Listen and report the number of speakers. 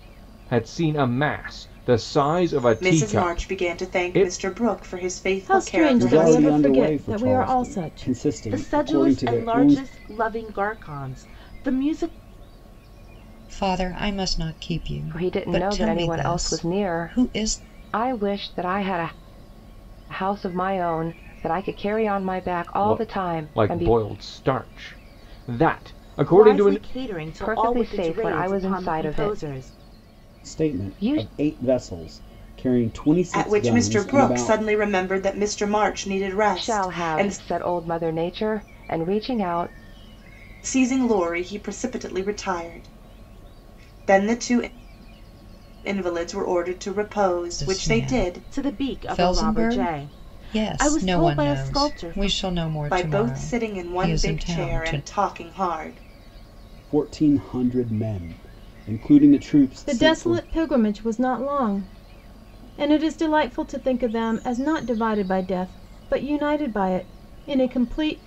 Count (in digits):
7